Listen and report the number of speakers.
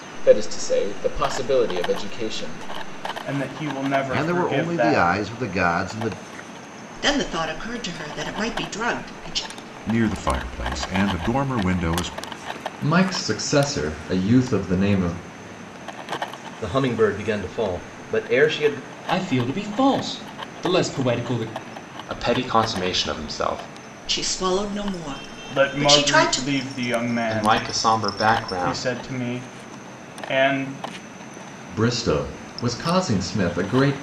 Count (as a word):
nine